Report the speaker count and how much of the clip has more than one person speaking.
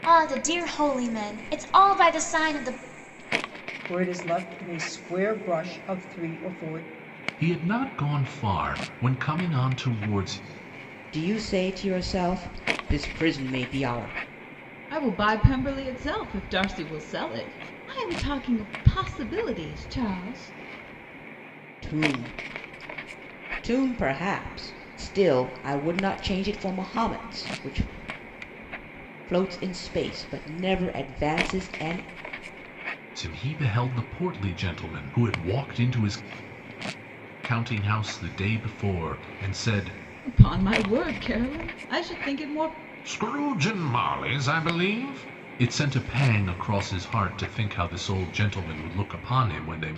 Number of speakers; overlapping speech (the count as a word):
five, no overlap